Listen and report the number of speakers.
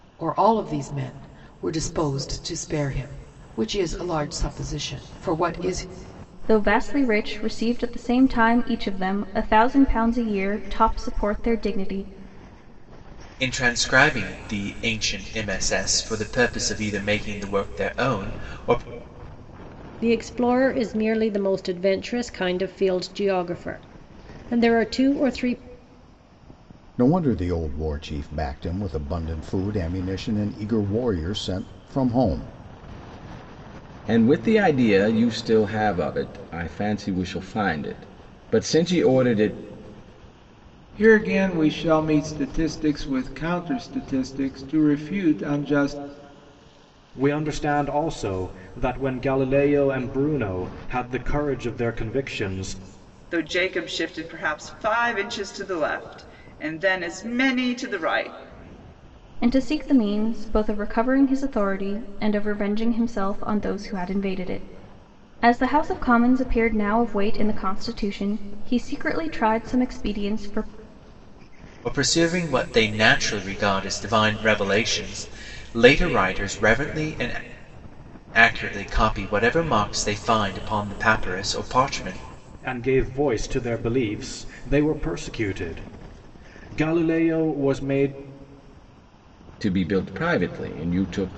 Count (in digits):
9